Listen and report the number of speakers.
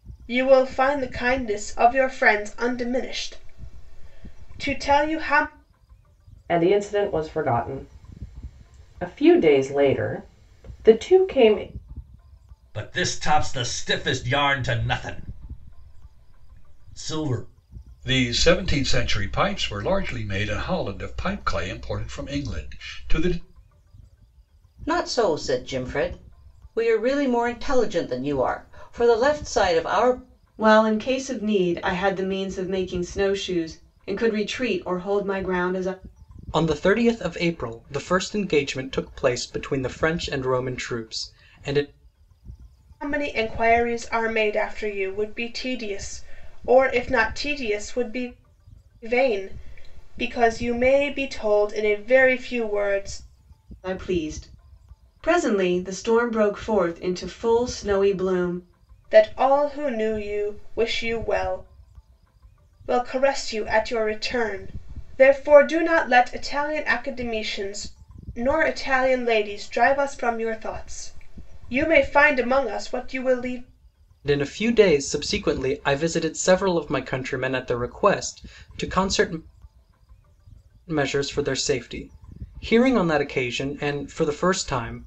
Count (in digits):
7